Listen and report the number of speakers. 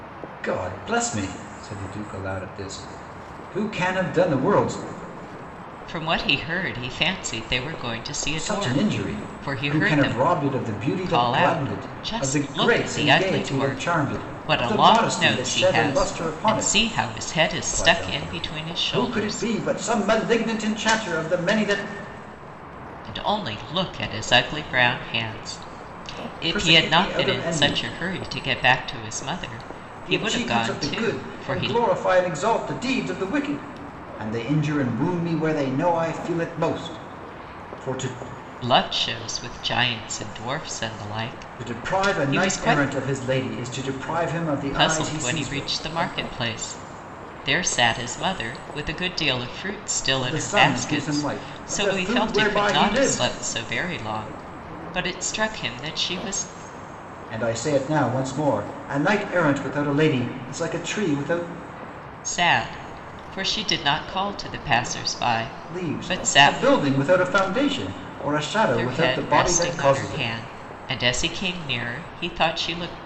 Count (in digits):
2